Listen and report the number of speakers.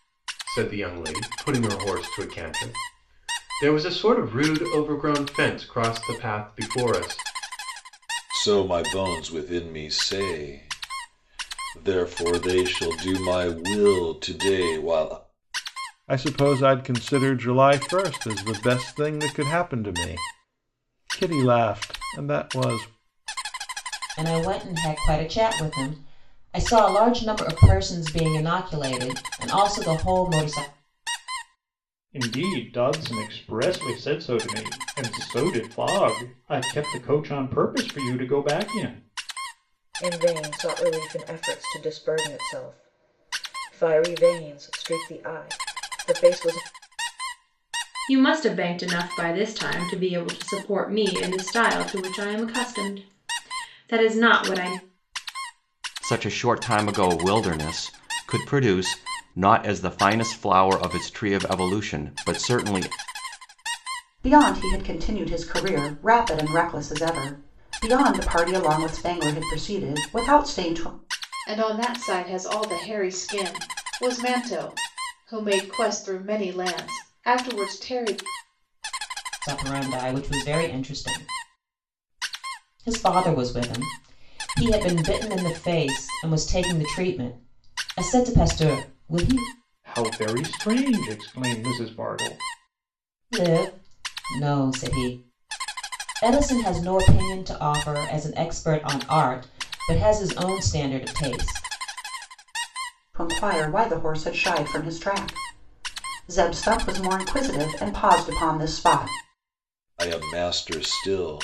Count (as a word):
ten